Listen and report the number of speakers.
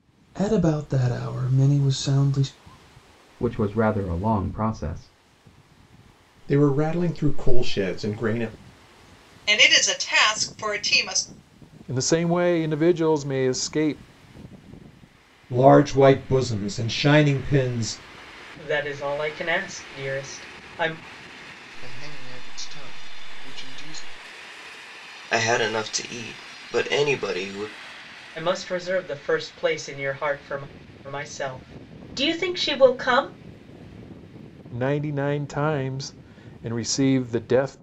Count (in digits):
9